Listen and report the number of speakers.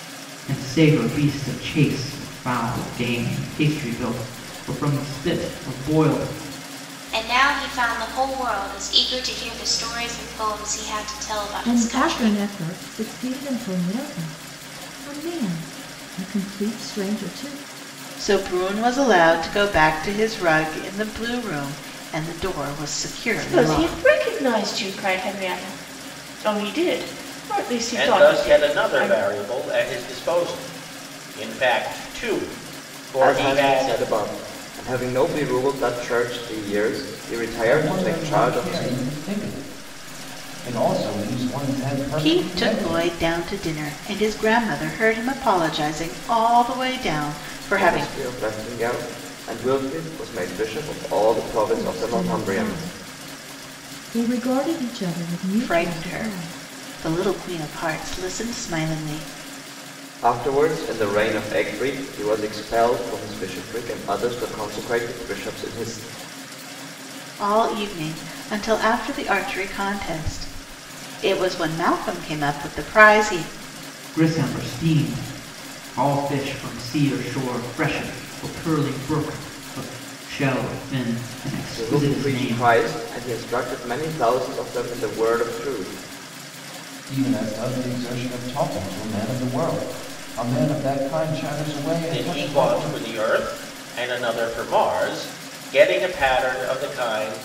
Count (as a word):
eight